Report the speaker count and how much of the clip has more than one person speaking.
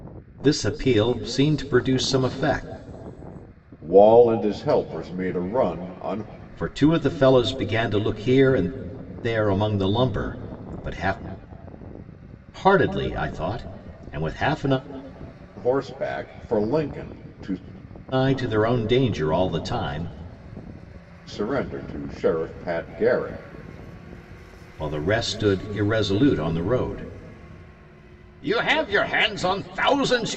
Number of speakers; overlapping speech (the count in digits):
2, no overlap